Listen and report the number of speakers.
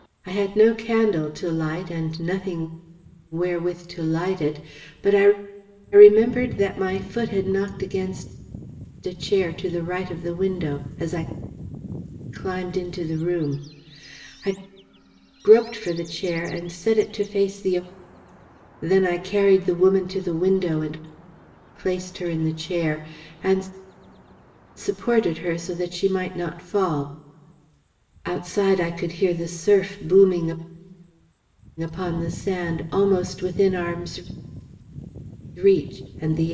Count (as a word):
one